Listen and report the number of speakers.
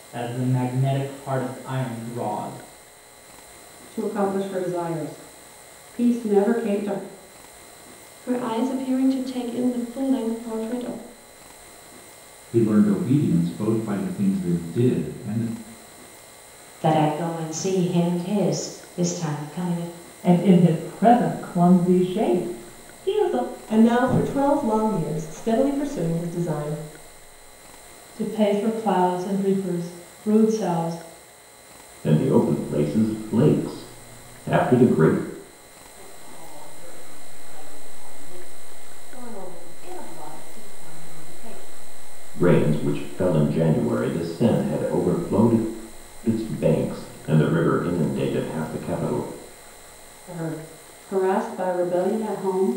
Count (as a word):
ten